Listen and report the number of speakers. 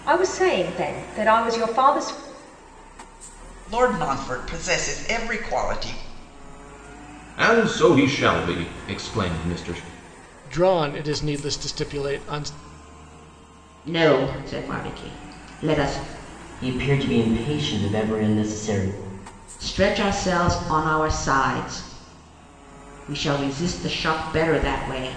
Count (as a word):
six